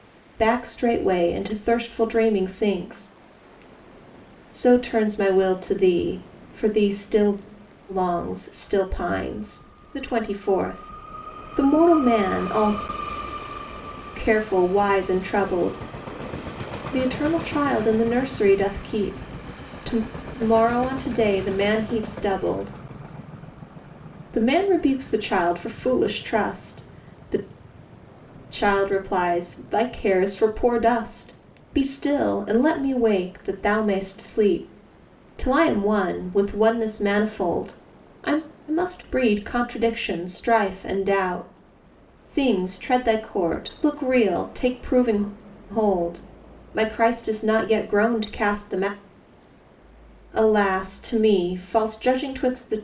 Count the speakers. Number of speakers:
1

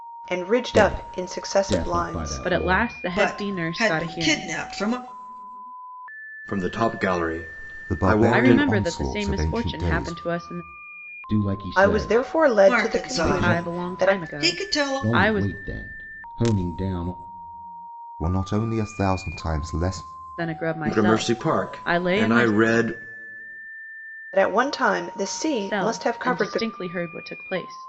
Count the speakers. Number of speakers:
6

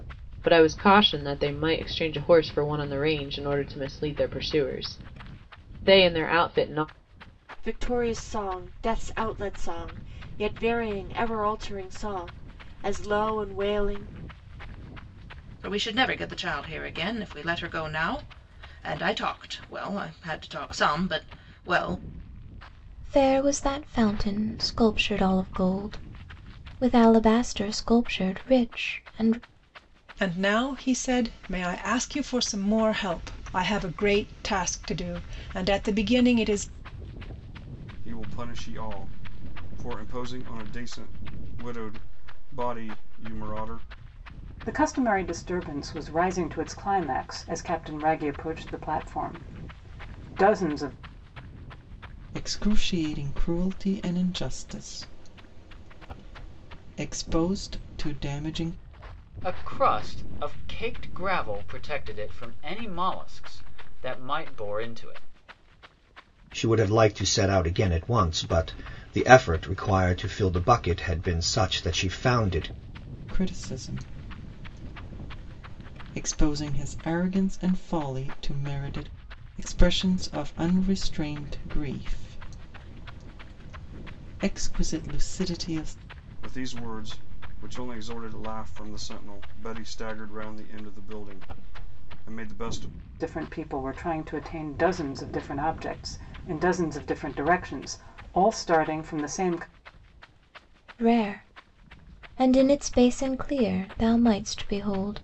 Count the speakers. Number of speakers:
10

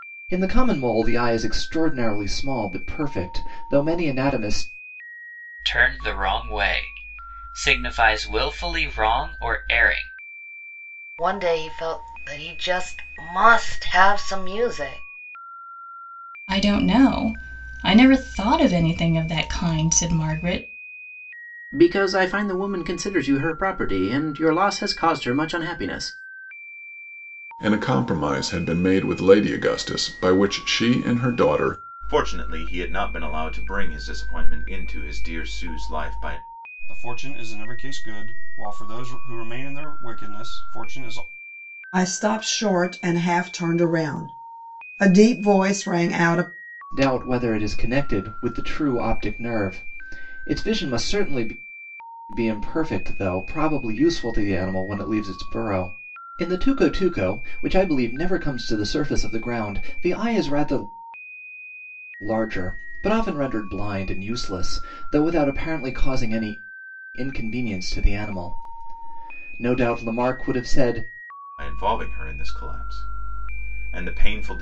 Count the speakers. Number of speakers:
9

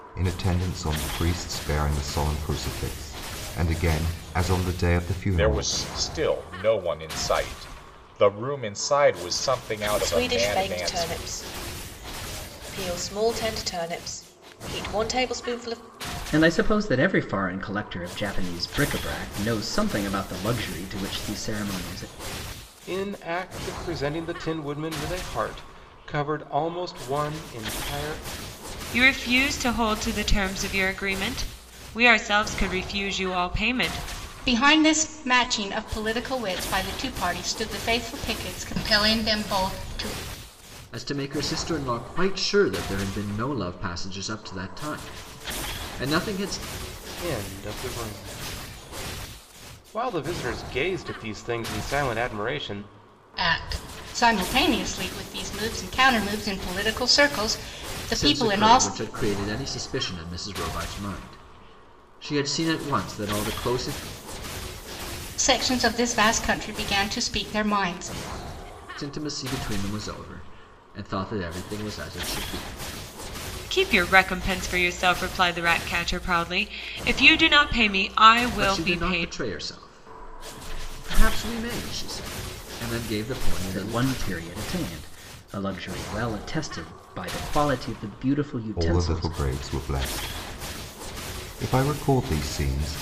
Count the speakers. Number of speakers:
8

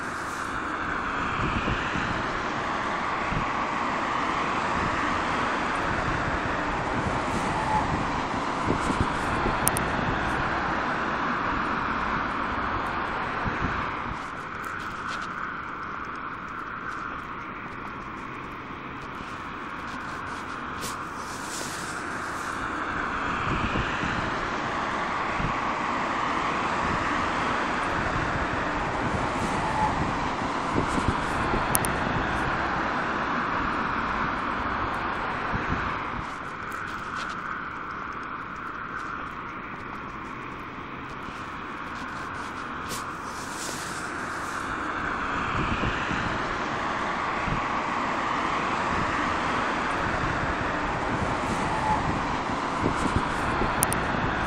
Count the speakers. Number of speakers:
0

